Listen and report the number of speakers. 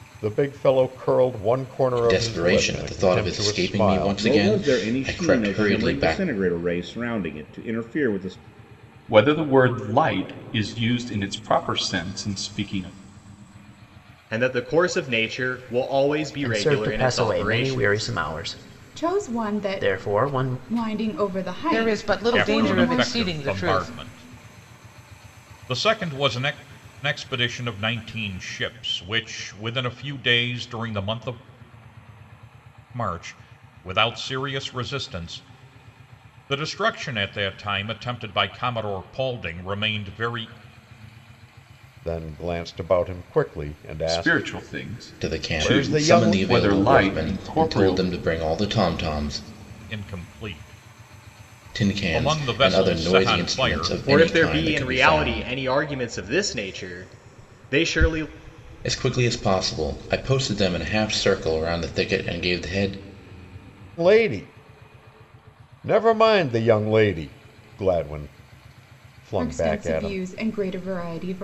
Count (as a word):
nine